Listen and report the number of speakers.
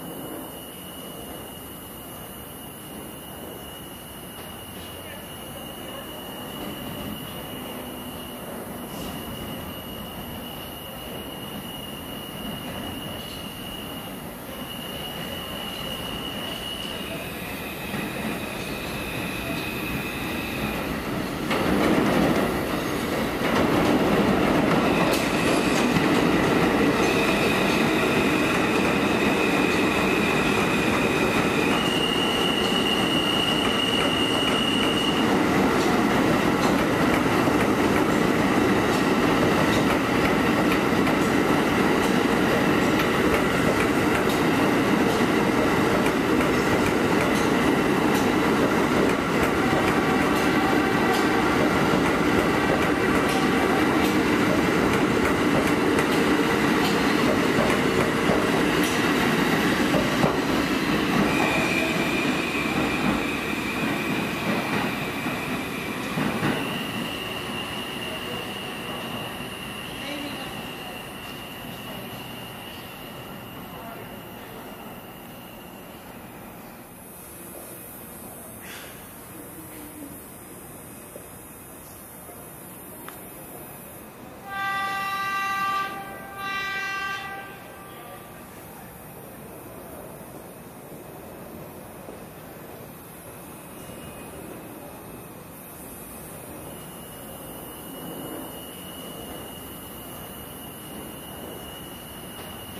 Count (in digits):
0